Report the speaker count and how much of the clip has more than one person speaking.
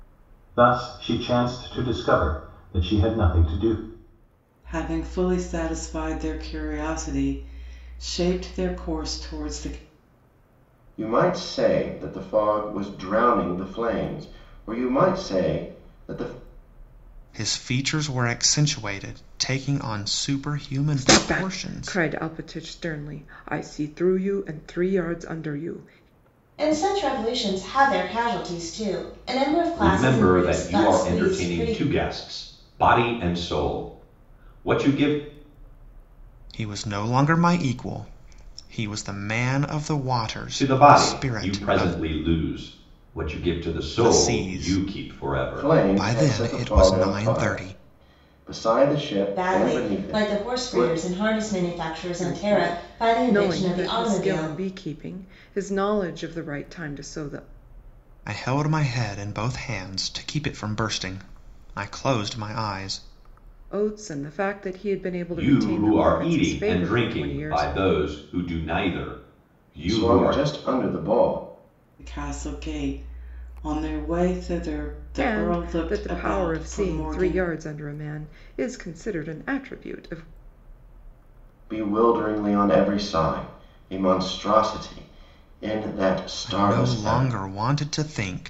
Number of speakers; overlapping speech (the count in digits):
7, about 21%